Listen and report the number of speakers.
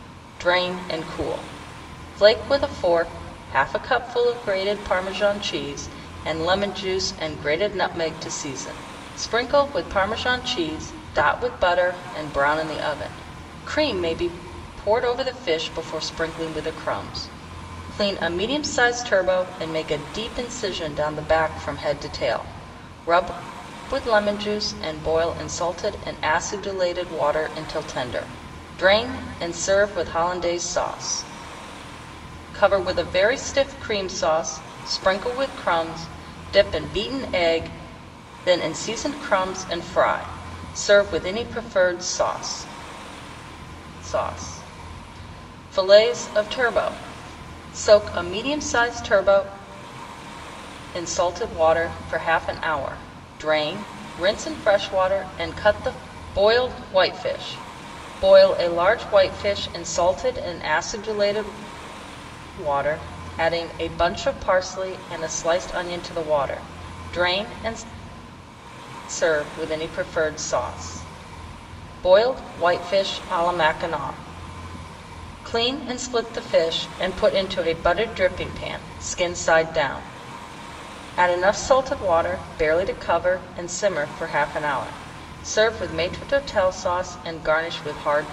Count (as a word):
one